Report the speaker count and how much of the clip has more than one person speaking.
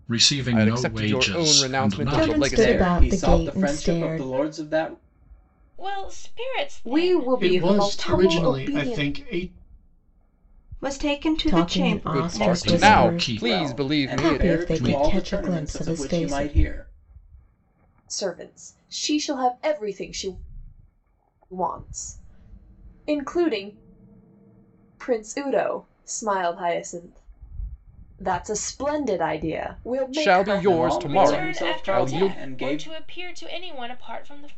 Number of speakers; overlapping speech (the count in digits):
8, about 41%